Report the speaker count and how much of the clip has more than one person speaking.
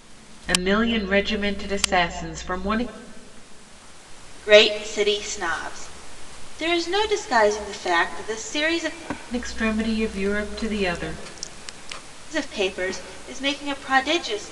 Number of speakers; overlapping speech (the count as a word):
two, no overlap